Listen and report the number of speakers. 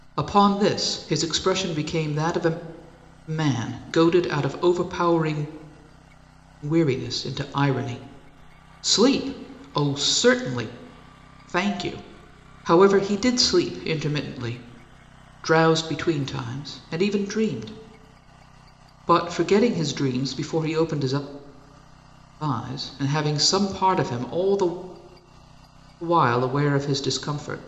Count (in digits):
1